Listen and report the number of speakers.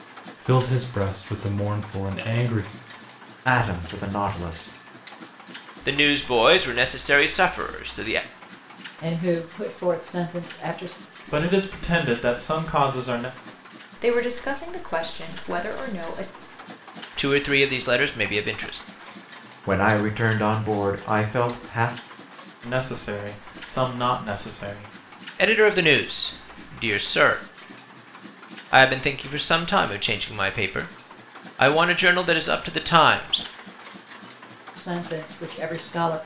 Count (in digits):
6